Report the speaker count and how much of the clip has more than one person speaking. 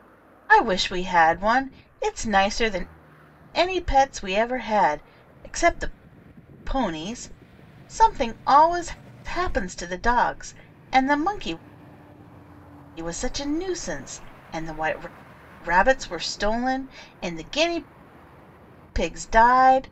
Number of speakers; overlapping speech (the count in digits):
1, no overlap